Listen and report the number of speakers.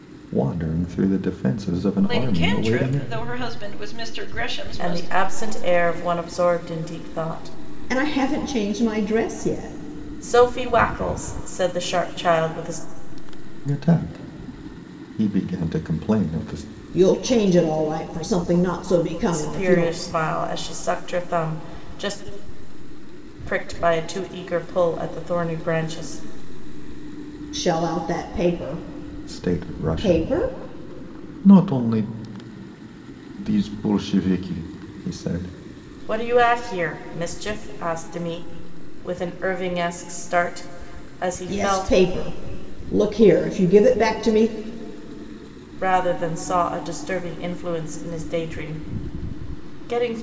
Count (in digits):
4